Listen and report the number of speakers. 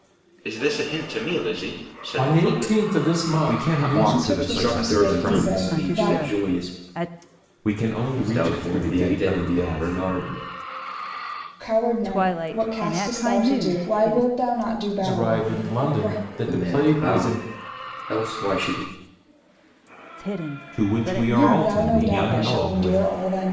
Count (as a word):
six